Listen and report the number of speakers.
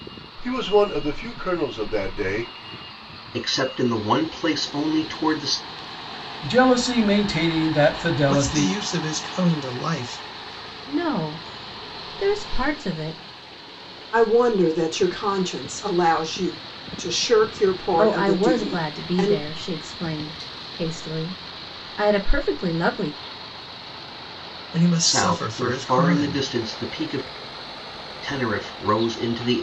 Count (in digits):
6